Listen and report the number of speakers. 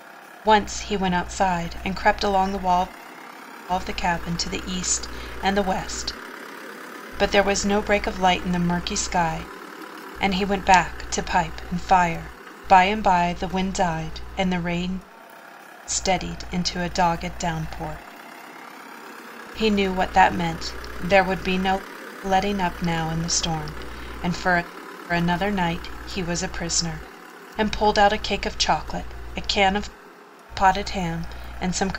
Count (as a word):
one